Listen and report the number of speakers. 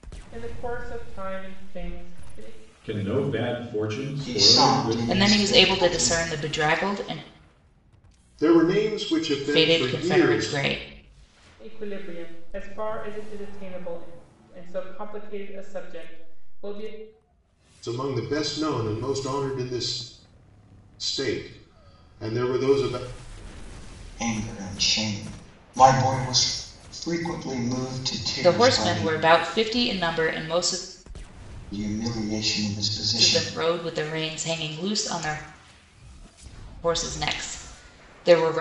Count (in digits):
5